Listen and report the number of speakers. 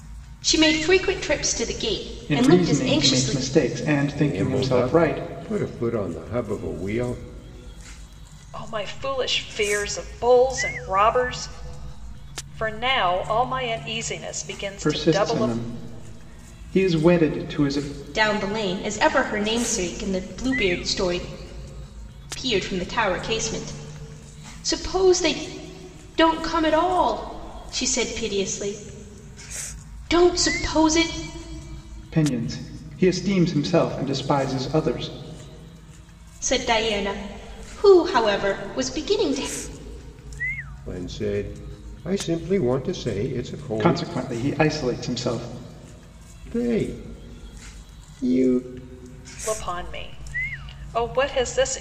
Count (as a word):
four